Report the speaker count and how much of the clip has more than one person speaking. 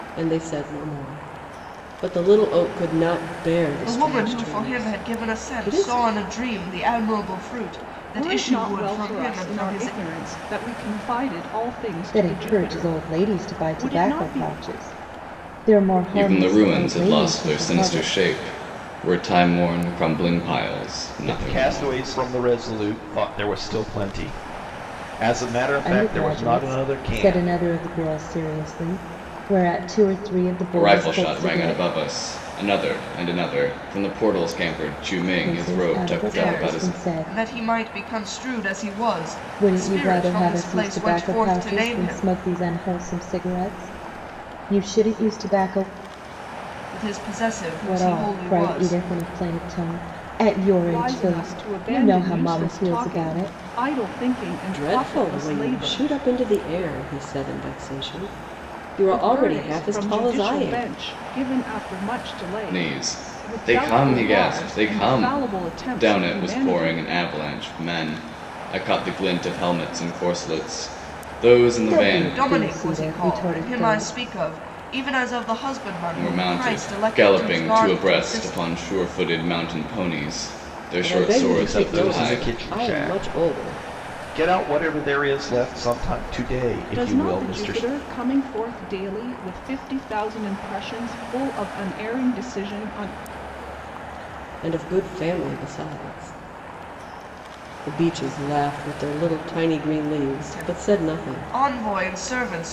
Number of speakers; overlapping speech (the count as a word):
six, about 37%